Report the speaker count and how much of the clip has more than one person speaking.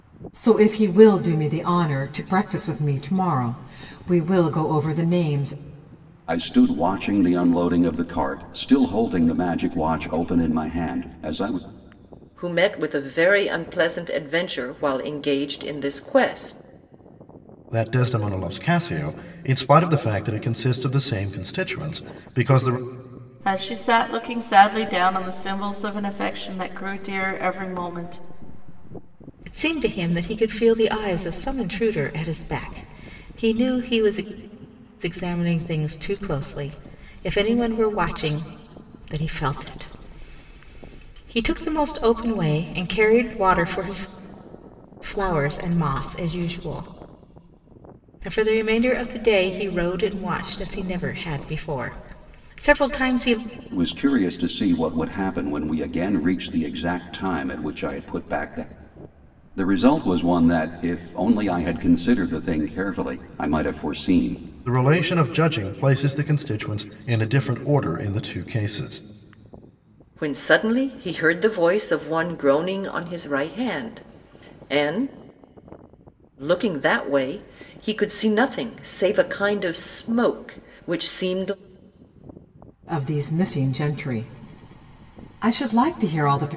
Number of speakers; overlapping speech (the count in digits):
6, no overlap